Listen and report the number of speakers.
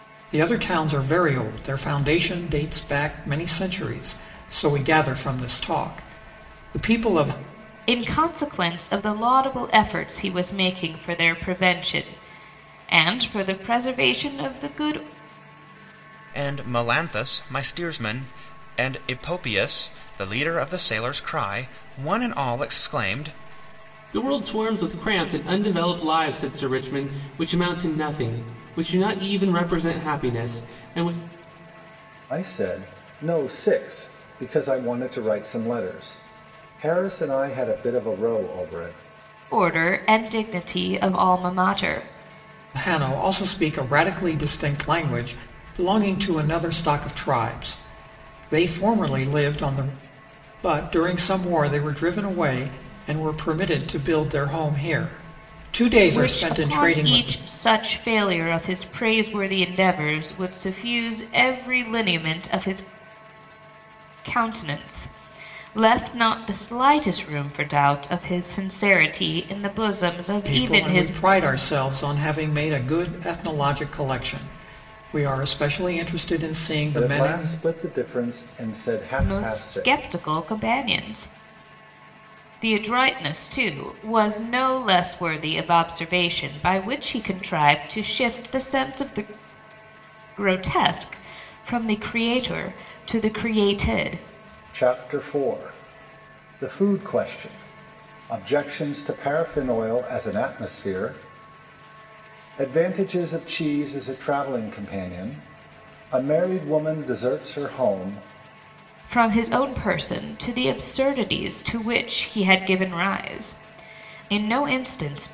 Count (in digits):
5